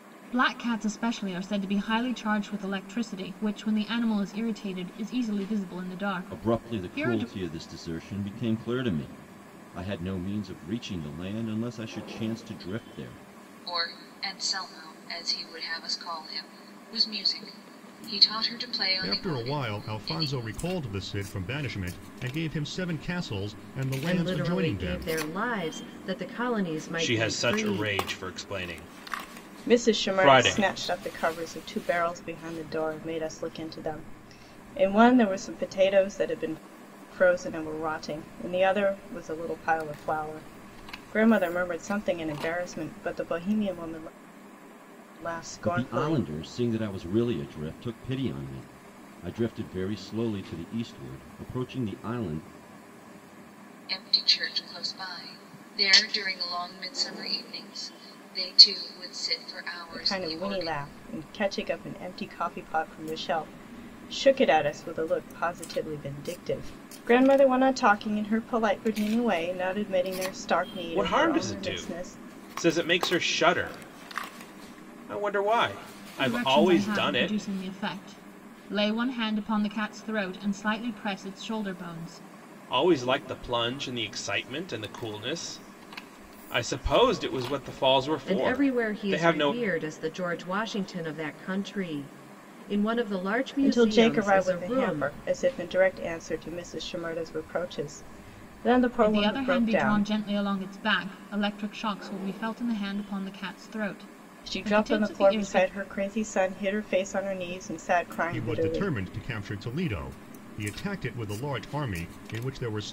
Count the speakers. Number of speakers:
seven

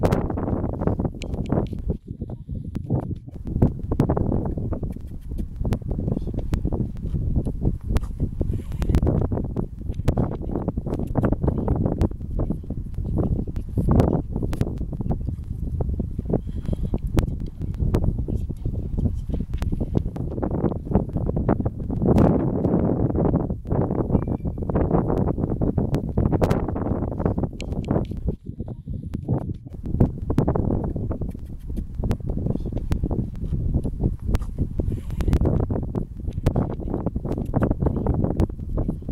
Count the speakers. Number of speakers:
zero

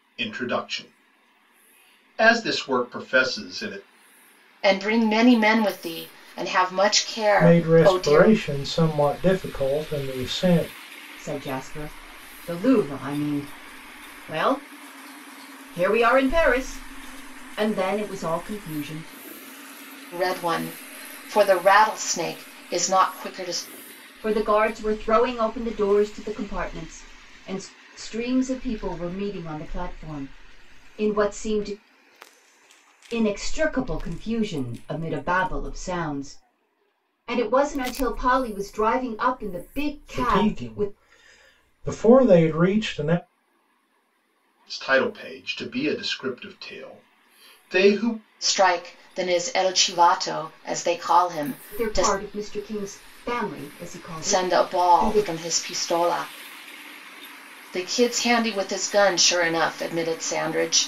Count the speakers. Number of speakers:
four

